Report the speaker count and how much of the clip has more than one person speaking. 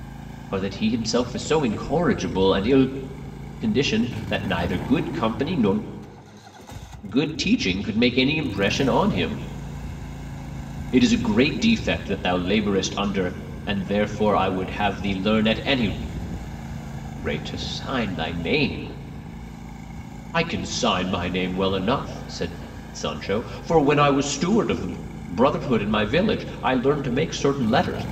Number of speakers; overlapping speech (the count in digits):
1, no overlap